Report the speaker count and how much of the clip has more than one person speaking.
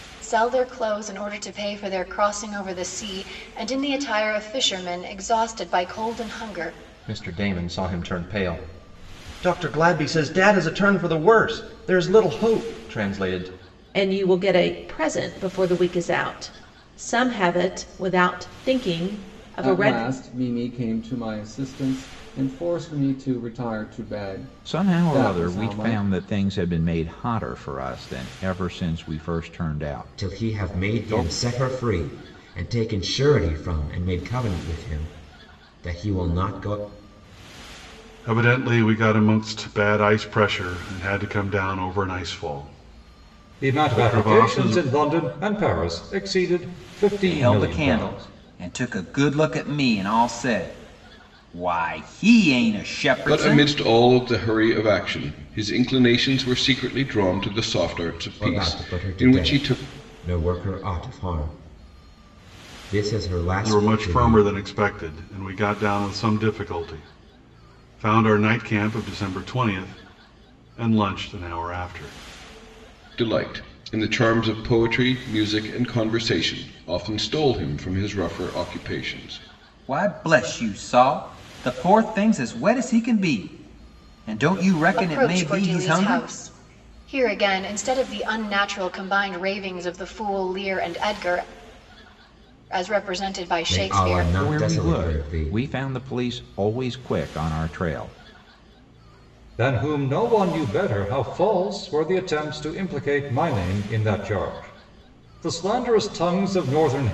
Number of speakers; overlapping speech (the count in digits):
10, about 11%